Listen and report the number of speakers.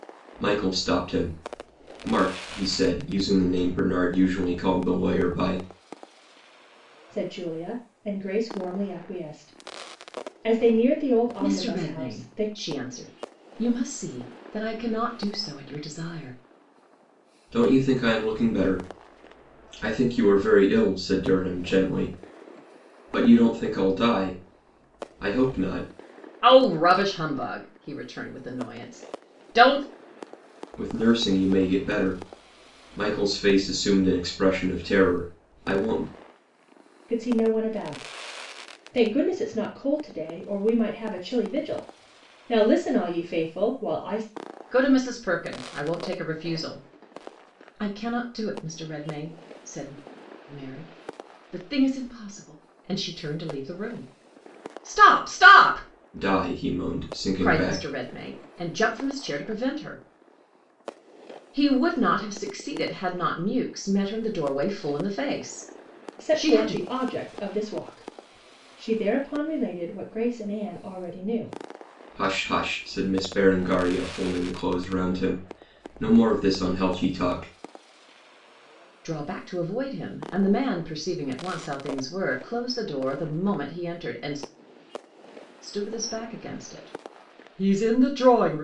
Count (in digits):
3